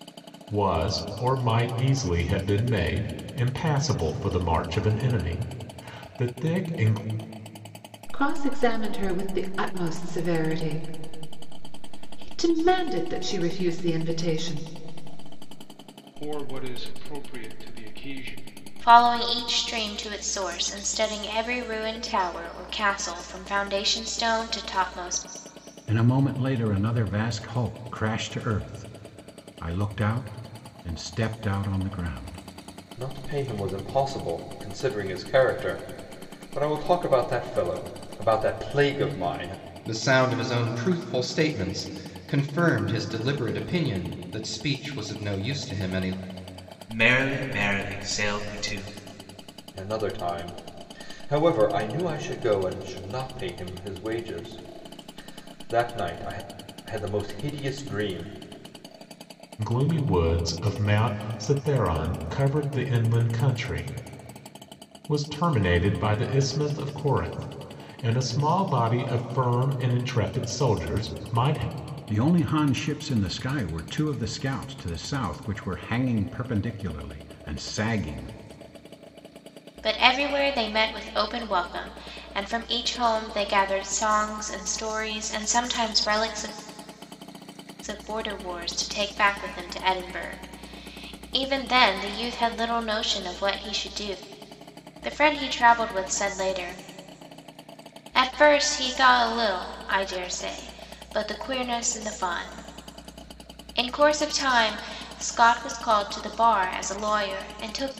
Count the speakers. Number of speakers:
eight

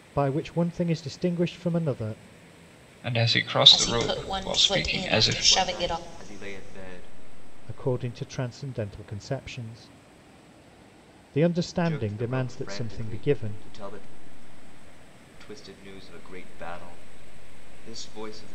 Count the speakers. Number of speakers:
four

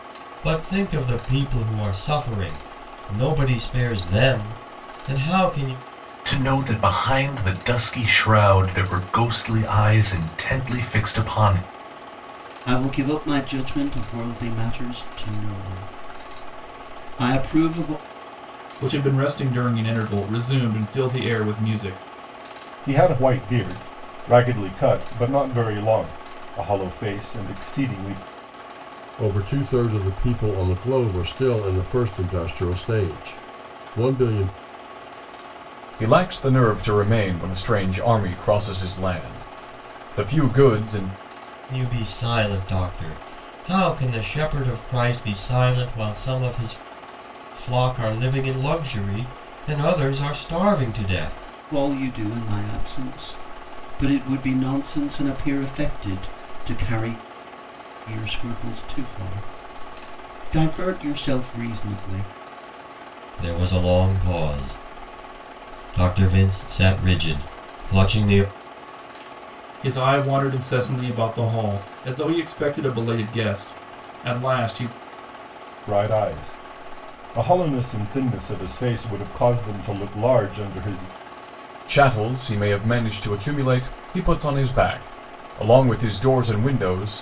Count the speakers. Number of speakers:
seven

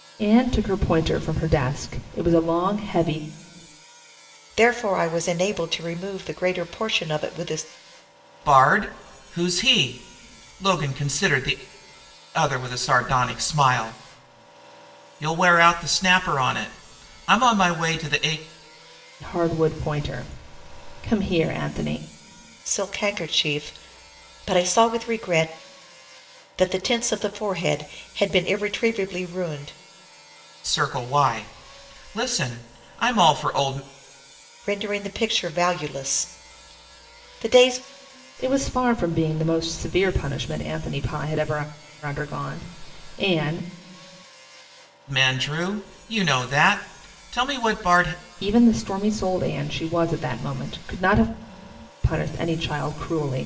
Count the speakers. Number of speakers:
three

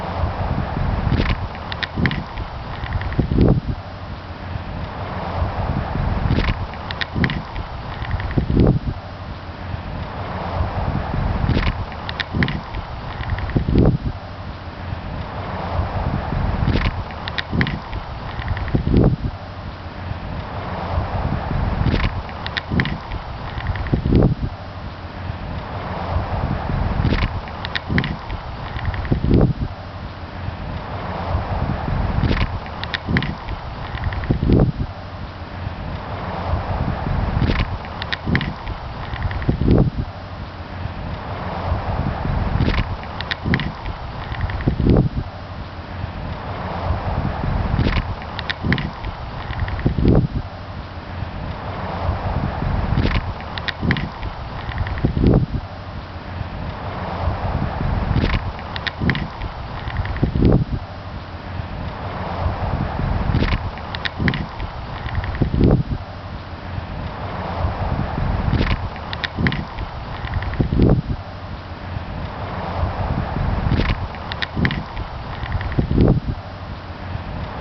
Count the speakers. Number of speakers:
zero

